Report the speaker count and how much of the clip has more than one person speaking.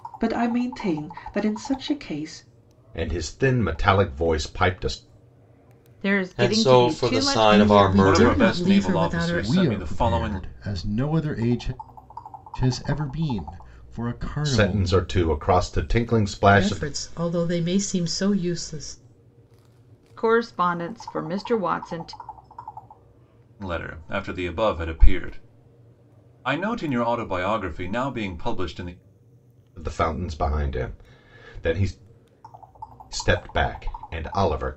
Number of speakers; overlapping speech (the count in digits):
7, about 14%